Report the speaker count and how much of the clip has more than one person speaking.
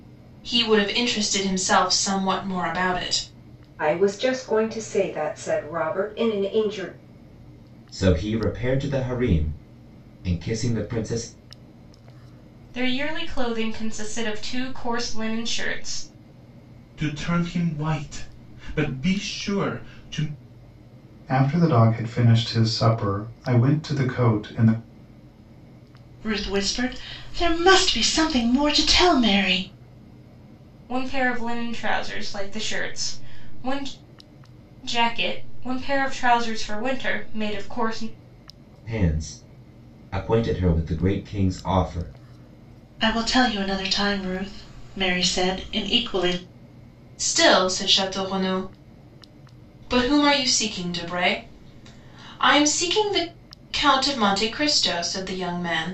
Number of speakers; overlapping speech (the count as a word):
seven, no overlap